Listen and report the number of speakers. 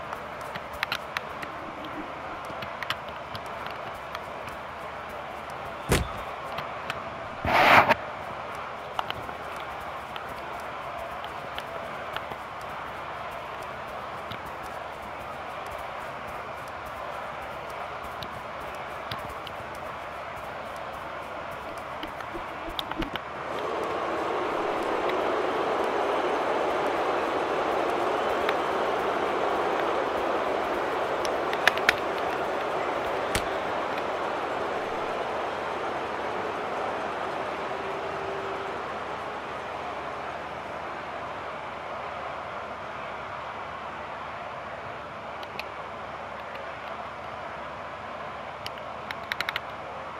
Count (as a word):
zero